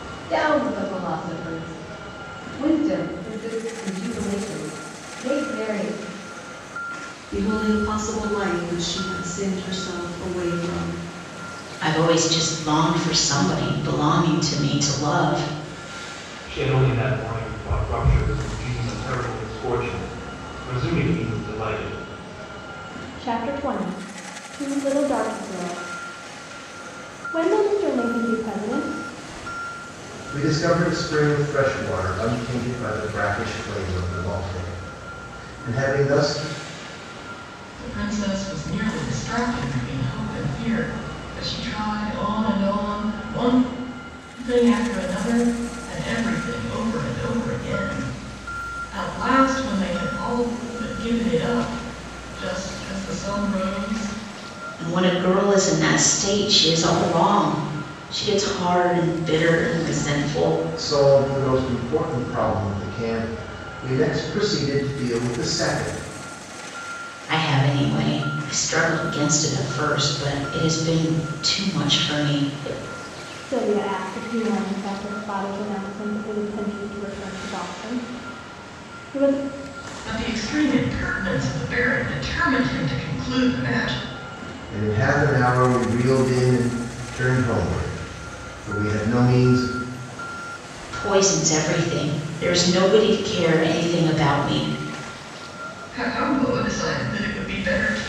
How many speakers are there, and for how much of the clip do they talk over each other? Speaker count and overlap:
7, no overlap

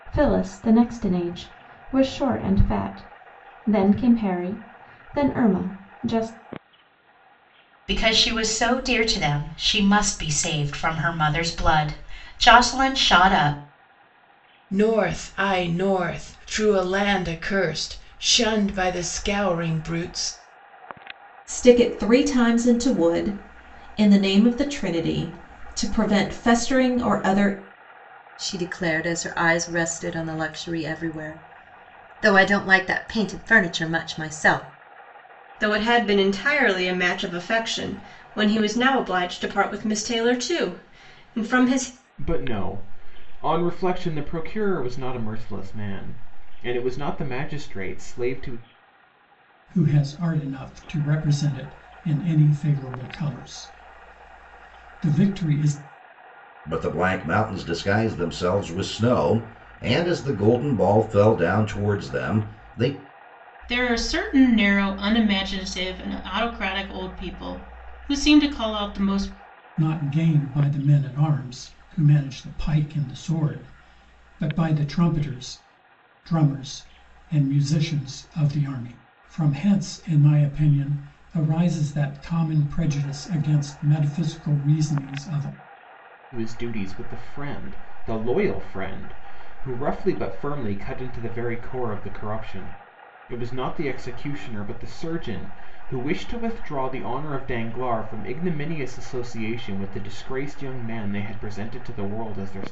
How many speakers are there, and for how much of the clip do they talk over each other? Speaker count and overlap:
10, no overlap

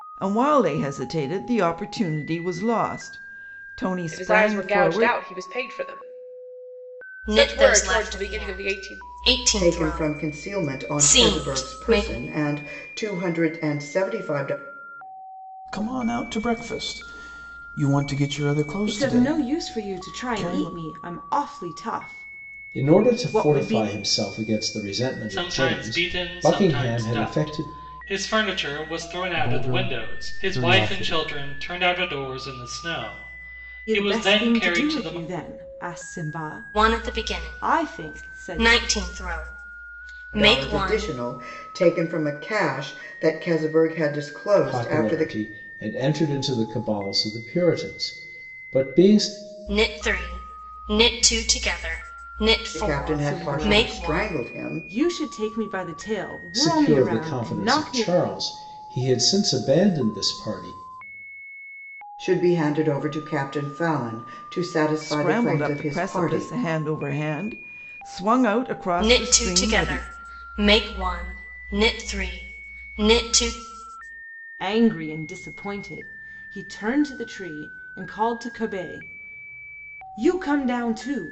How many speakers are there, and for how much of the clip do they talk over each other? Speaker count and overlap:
9, about 30%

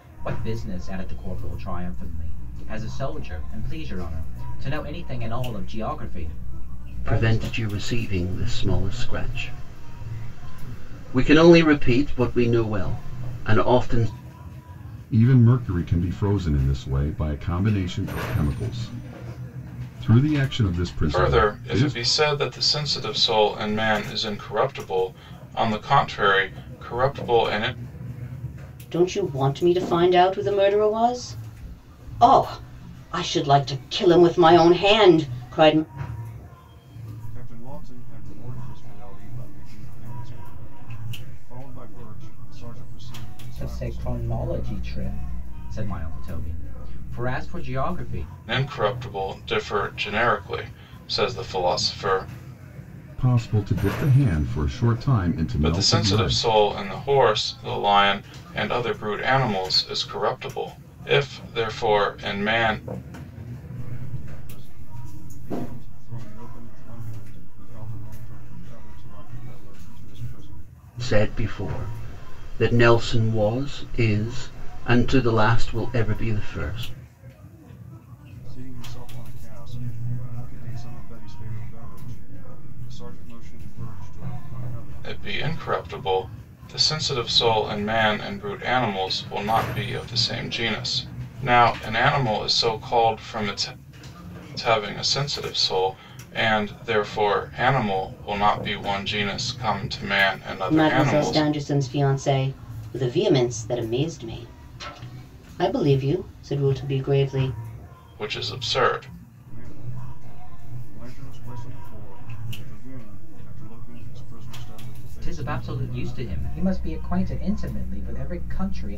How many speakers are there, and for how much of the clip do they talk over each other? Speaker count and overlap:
6, about 5%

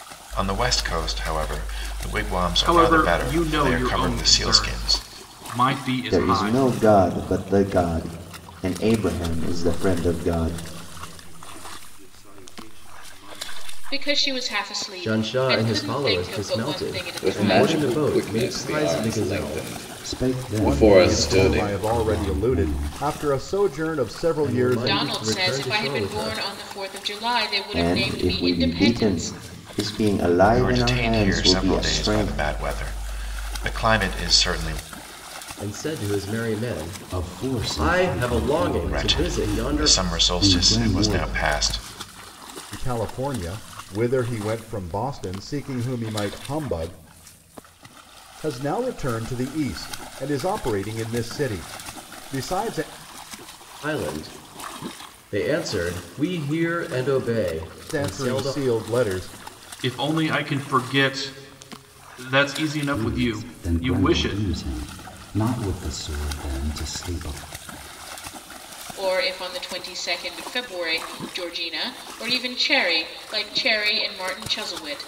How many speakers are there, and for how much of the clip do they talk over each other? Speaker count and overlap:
9, about 32%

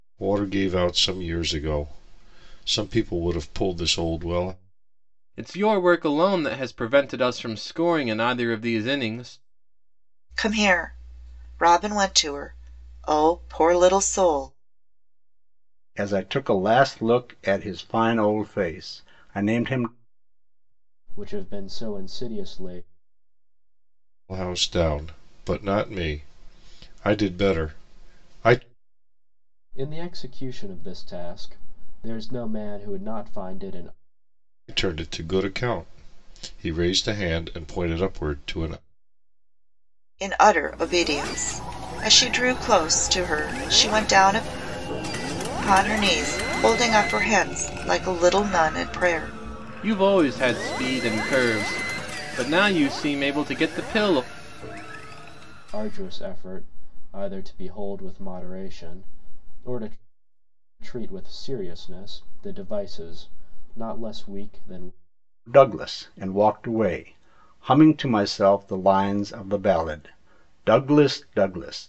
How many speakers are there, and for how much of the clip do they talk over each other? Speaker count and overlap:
5, no overlap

